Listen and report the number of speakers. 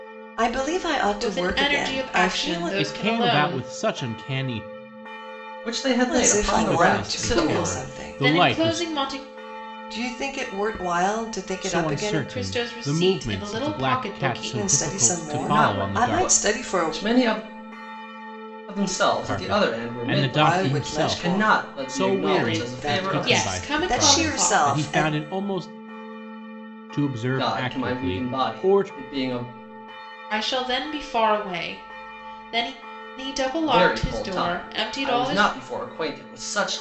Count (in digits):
4